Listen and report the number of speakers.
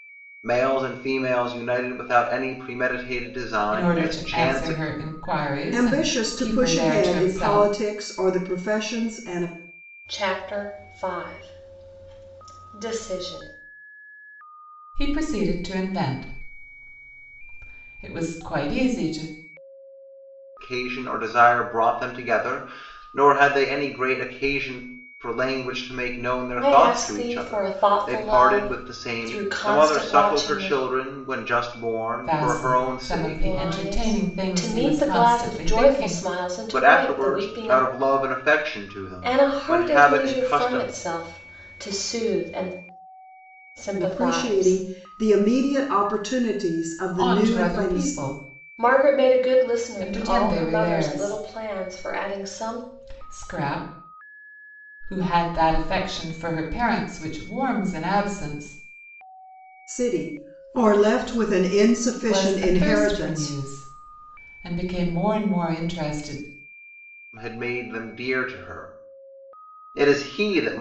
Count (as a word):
four